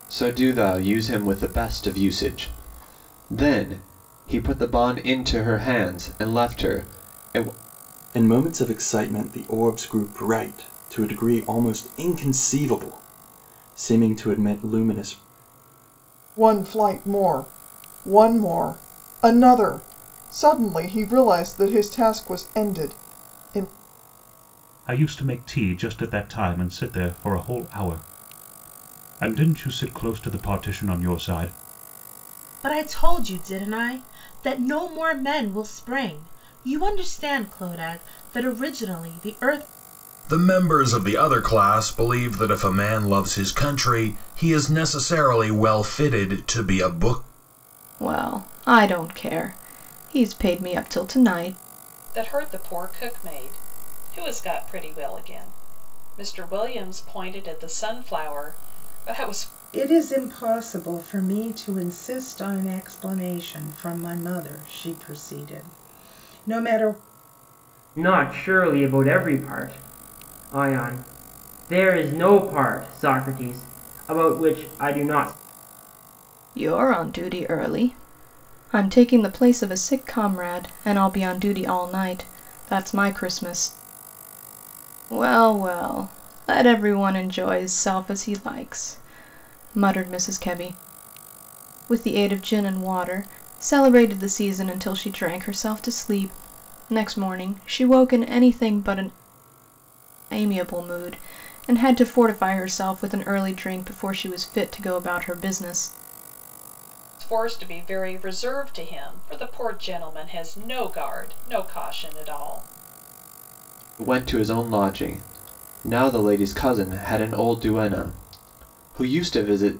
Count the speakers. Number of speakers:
ten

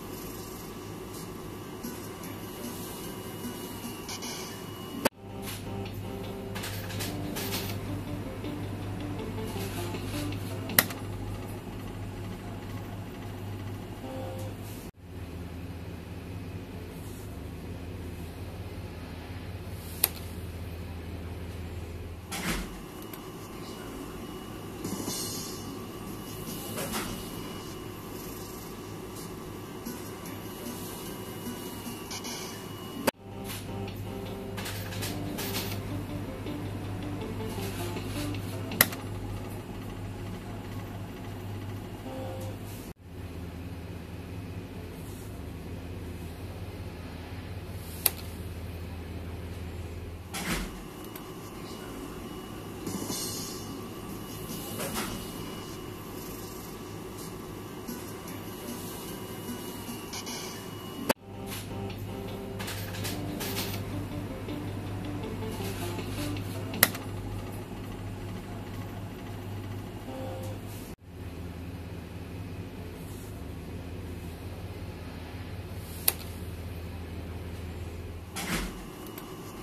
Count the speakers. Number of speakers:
zero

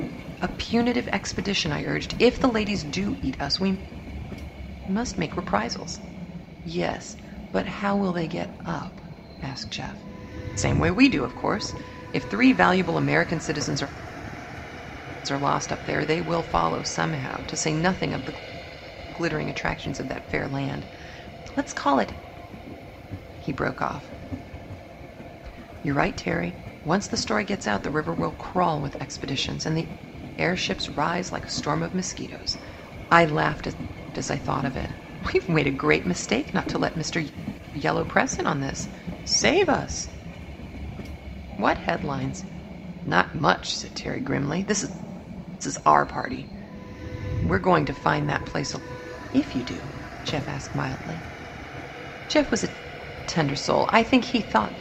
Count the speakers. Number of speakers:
one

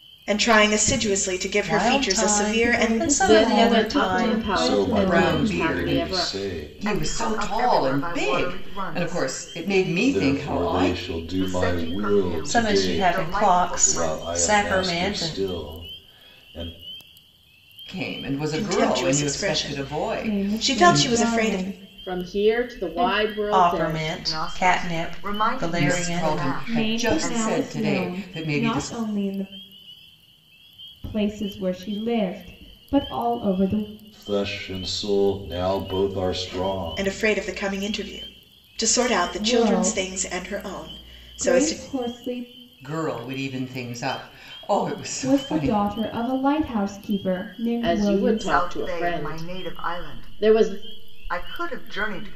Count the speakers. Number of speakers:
seven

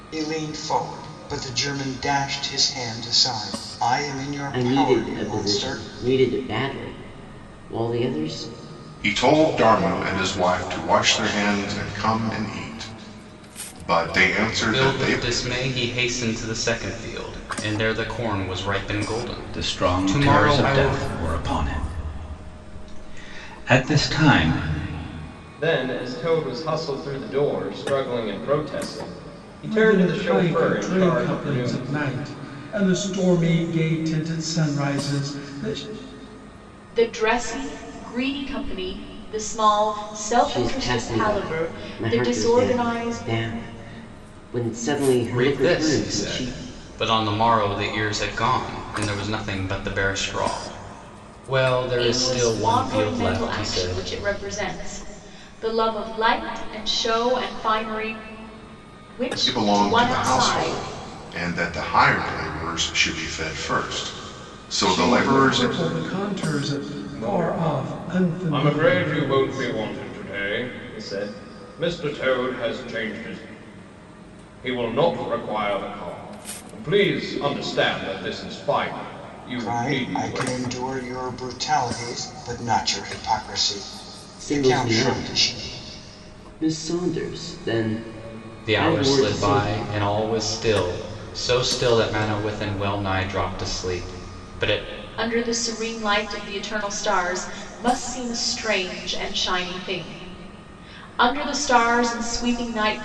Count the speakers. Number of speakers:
eight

